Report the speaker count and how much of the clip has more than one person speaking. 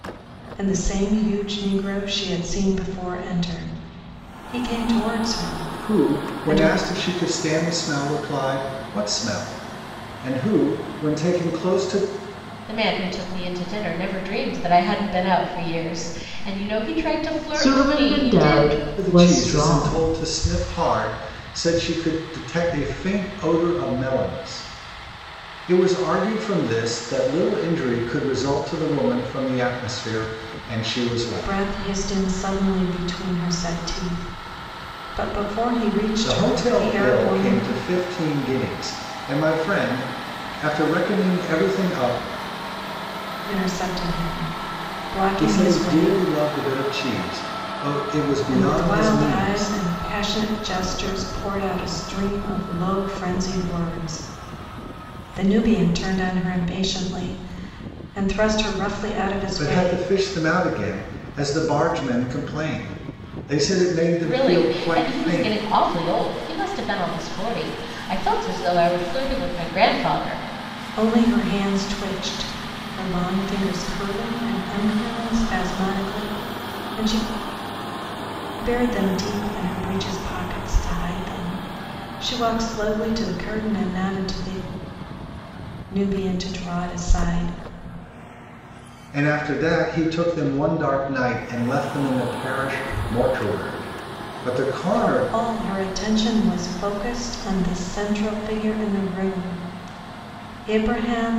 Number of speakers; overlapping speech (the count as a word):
four, about 9%